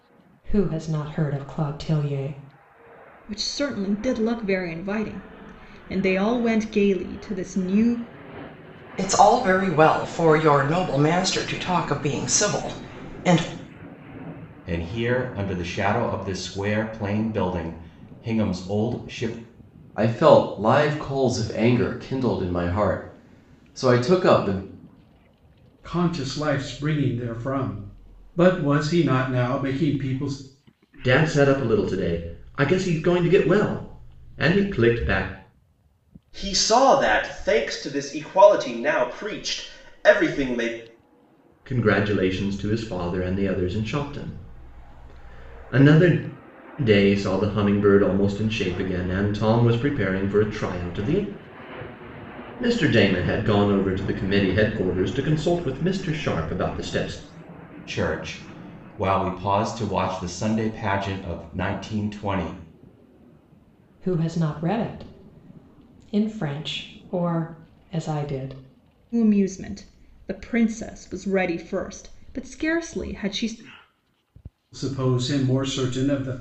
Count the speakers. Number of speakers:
8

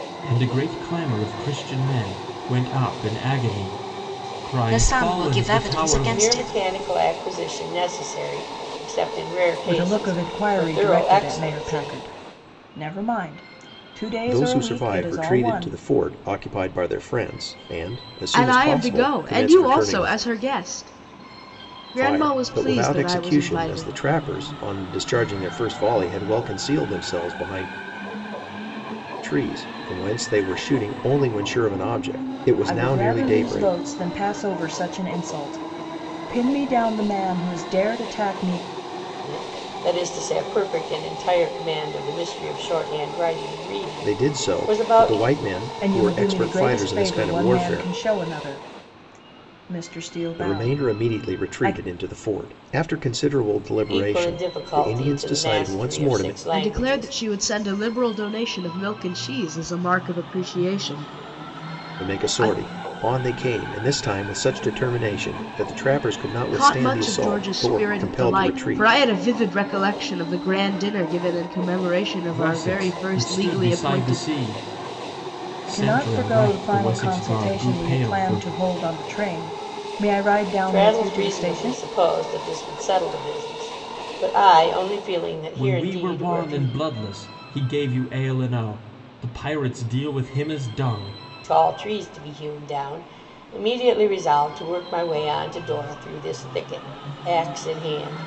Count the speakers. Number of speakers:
6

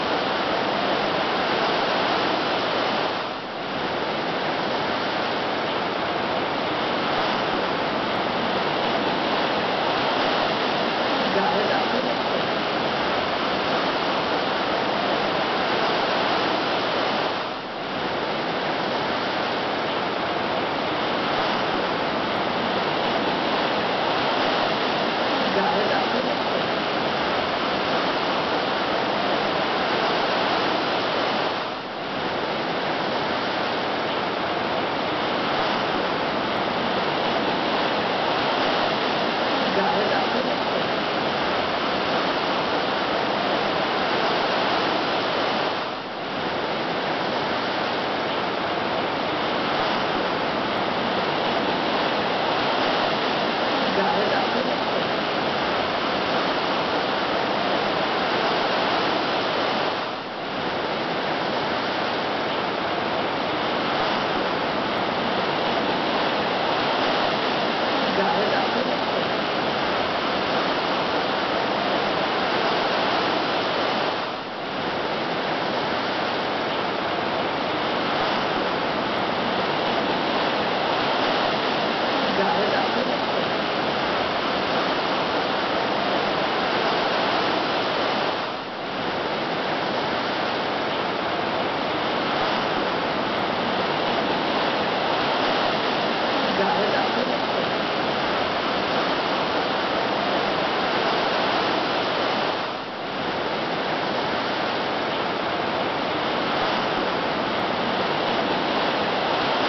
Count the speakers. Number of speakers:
0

